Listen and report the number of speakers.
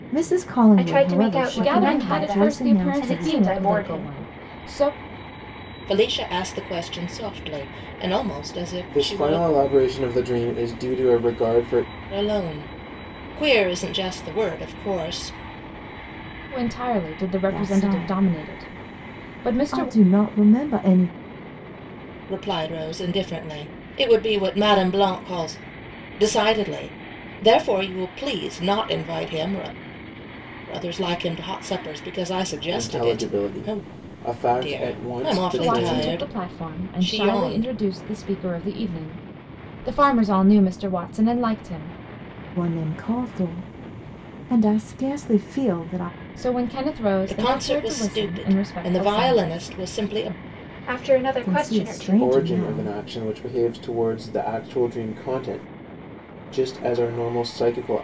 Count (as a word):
five